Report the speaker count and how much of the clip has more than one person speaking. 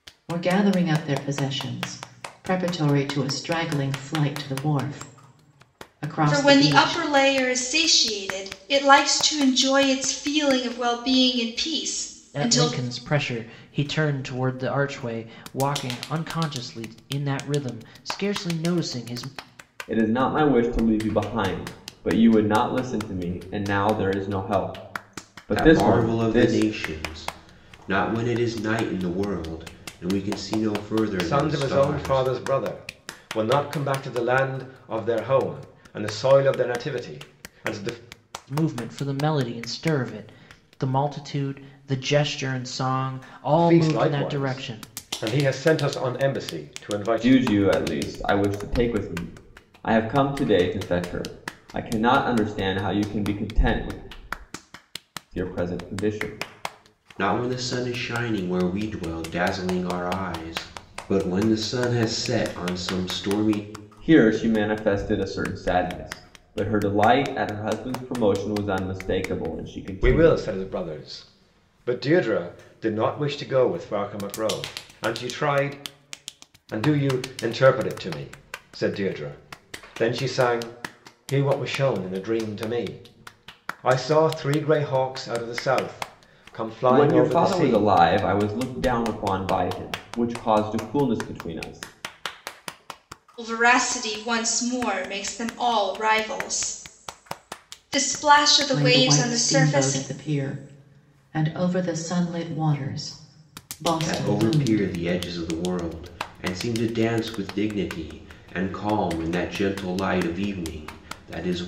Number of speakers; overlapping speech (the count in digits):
6, about 8%